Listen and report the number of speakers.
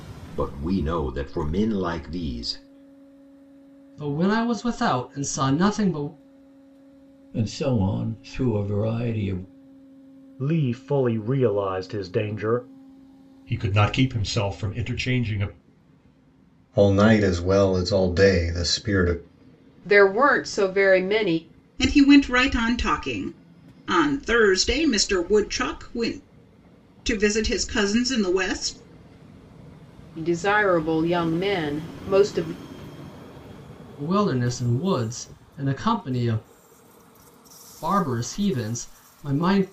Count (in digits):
8